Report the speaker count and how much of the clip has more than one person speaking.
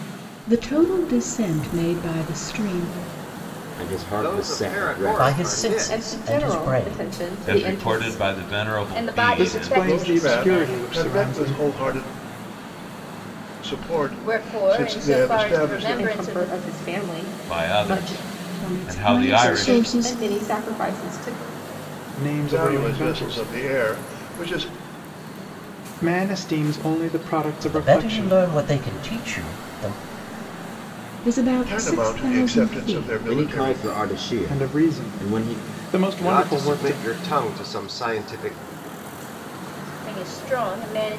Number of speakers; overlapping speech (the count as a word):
nine, about 42%